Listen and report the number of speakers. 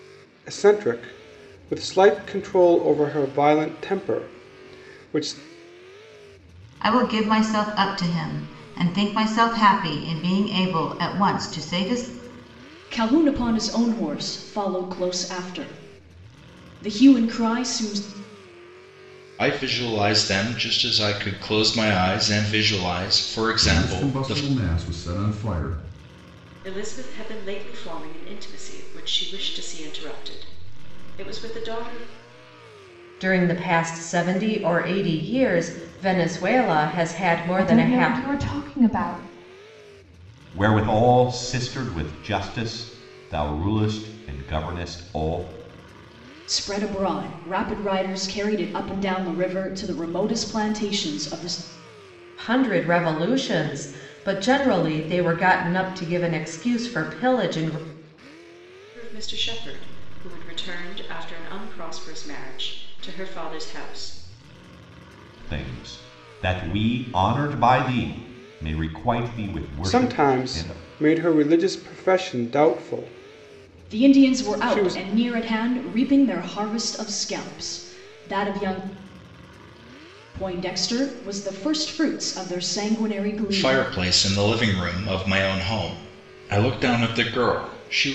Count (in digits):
9